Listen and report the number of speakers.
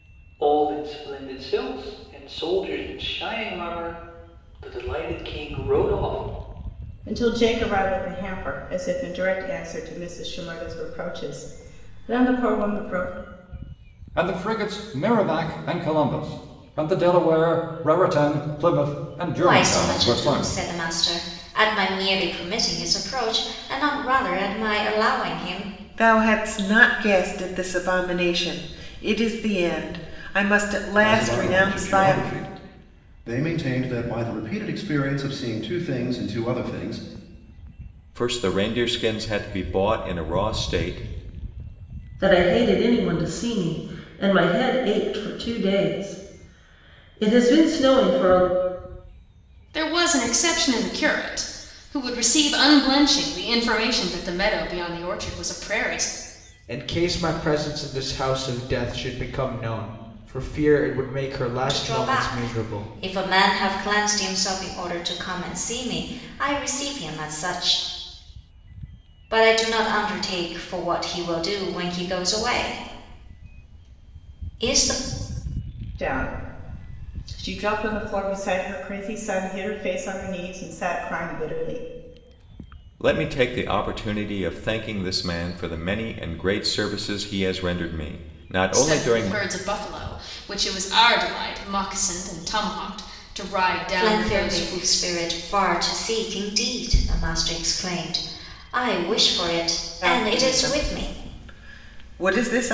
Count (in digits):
10